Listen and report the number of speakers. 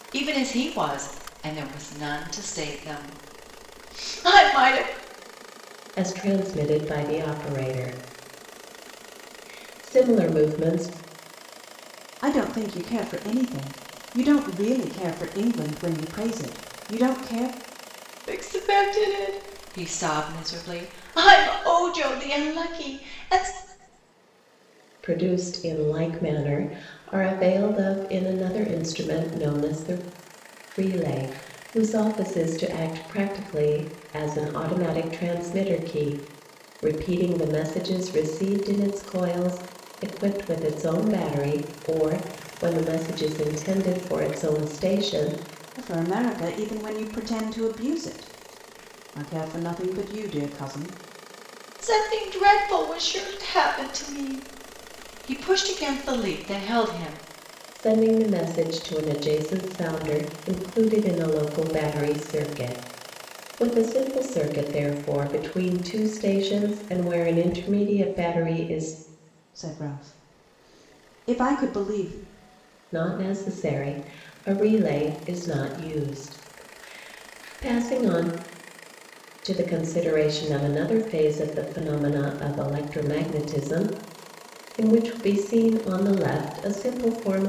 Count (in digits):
3